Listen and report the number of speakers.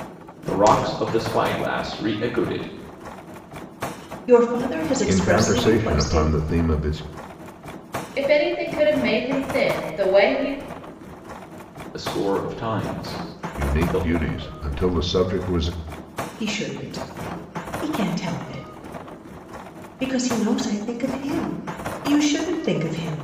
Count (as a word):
four